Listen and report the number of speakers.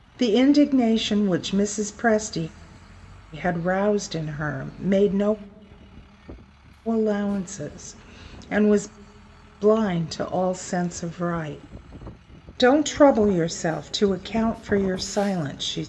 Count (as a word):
one